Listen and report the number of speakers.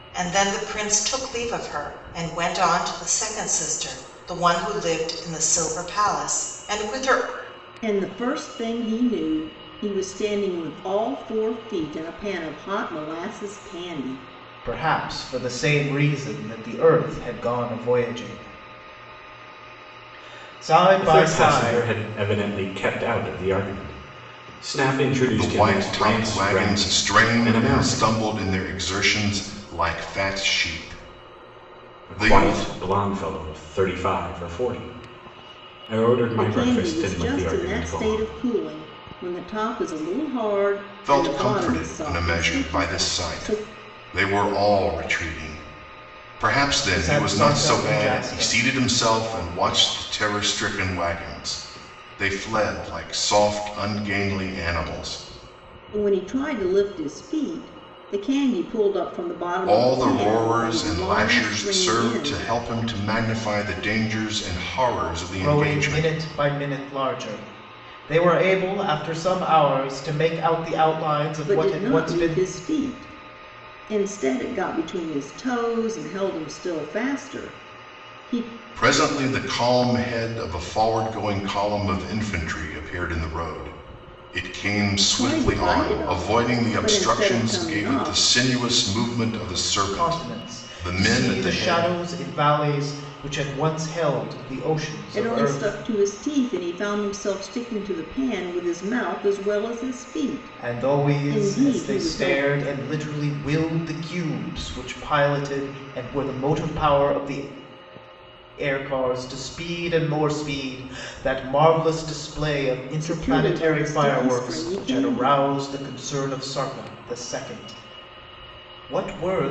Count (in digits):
5